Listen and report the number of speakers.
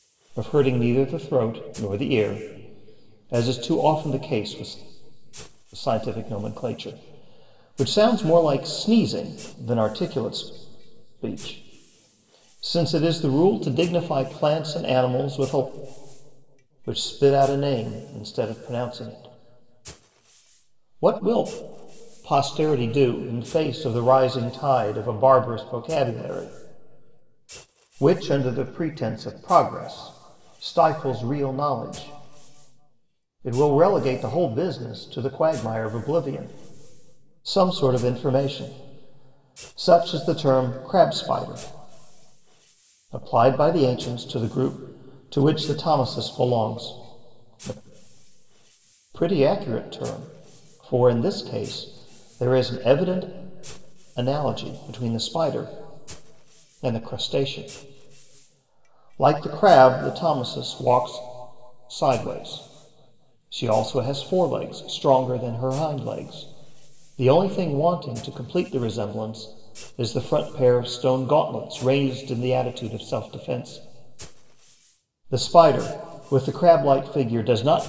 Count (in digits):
1